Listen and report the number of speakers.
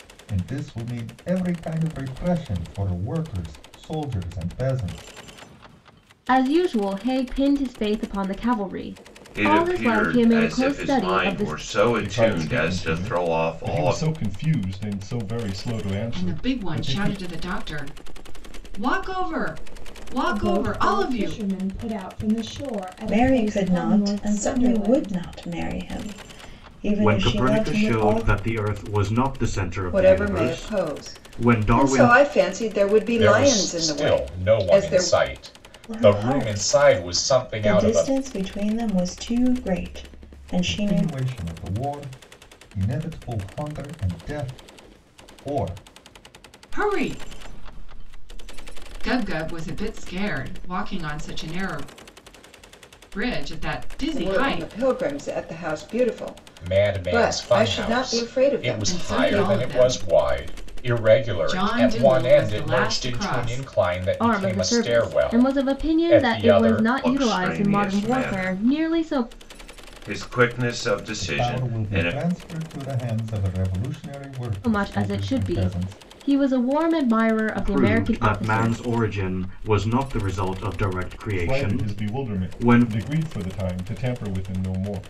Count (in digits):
10